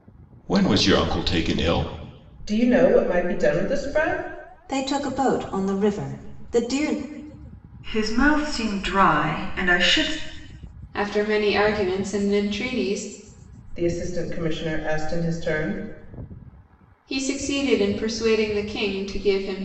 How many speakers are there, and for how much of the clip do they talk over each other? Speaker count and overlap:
5, no overlap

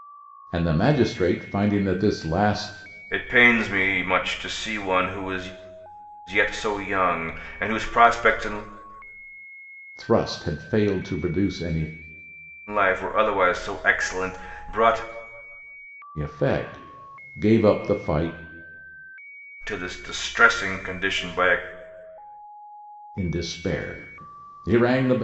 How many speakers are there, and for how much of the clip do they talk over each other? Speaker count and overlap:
2, no overlap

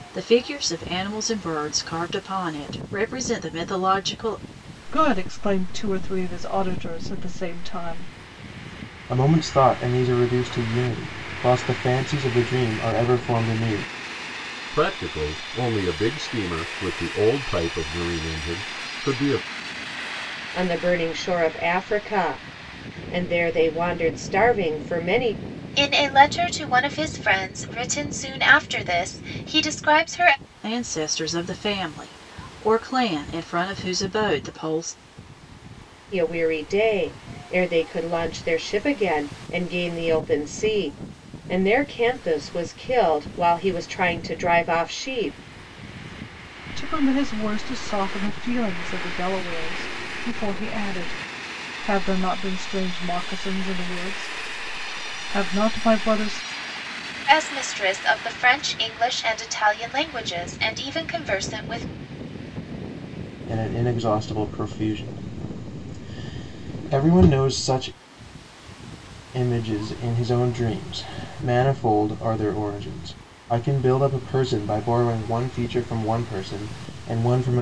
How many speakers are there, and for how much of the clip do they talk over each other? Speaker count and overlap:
6, no overlap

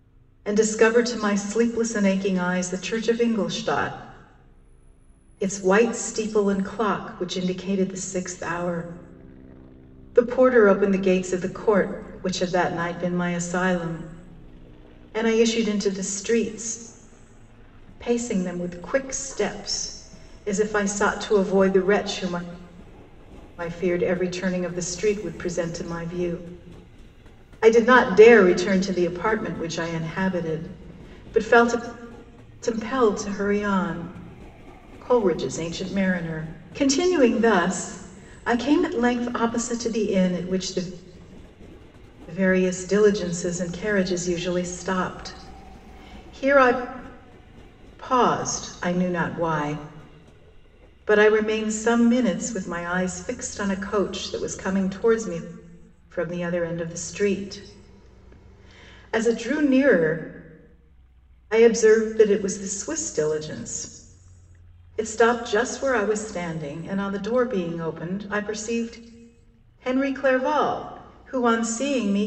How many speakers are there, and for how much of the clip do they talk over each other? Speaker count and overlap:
1, no overlap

